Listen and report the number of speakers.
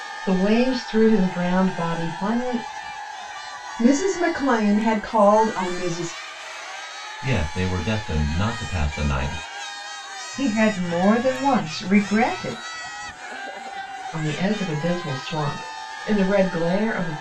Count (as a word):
four